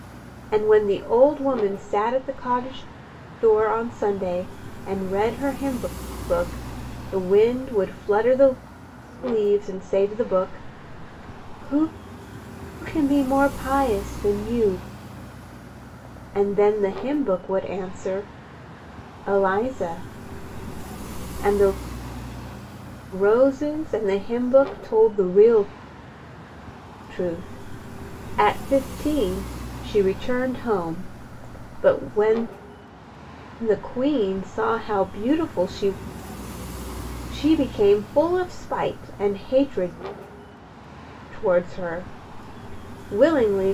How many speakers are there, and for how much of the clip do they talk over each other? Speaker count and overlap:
1, no overlap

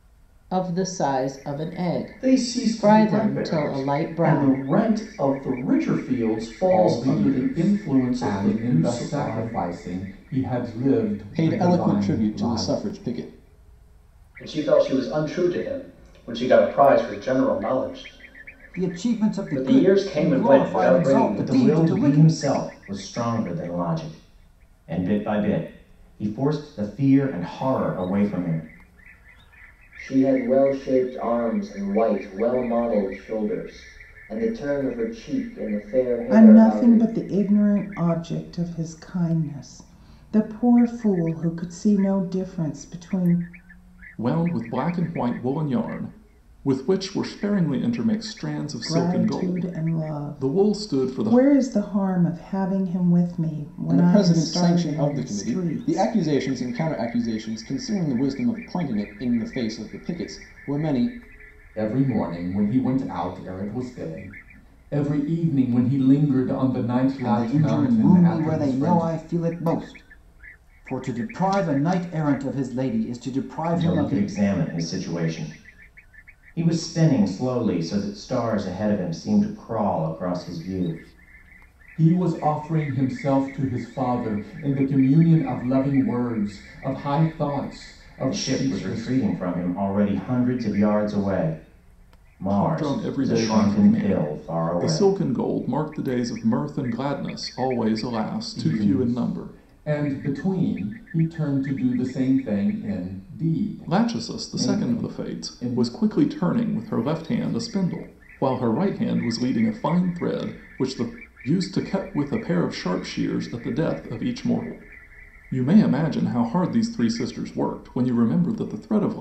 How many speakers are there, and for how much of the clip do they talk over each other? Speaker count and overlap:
10, about 22%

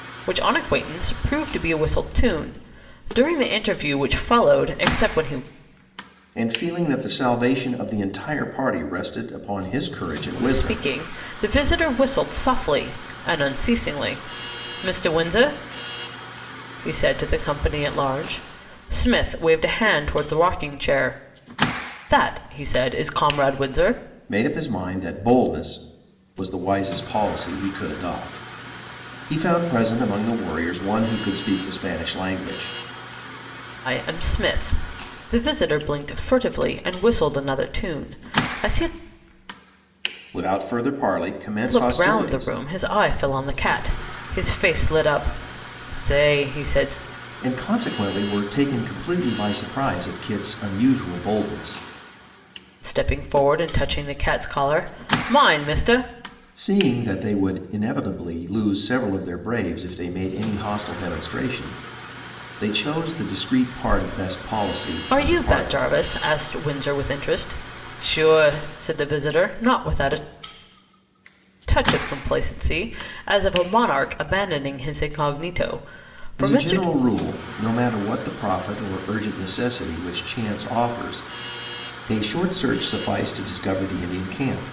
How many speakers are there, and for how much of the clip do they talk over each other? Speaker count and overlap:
2, about 3%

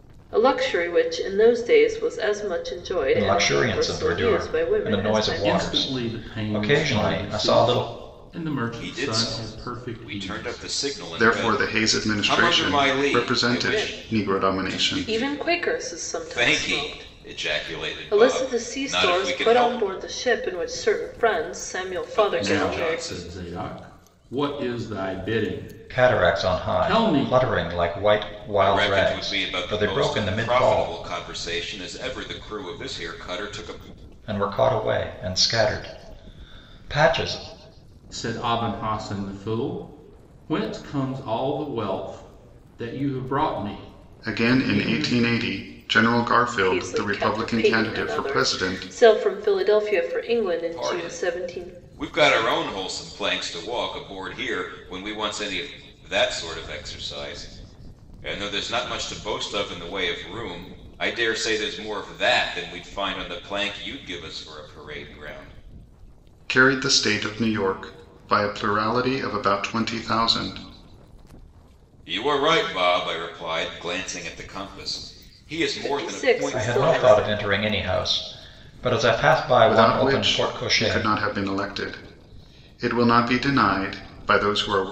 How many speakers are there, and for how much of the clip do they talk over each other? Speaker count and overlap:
5, about 32%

